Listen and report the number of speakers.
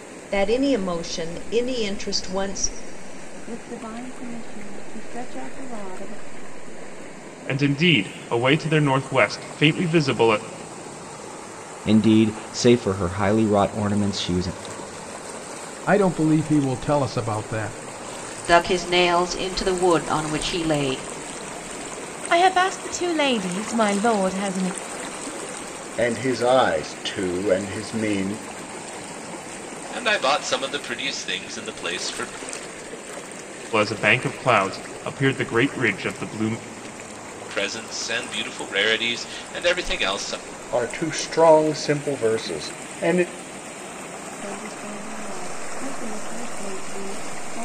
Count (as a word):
nine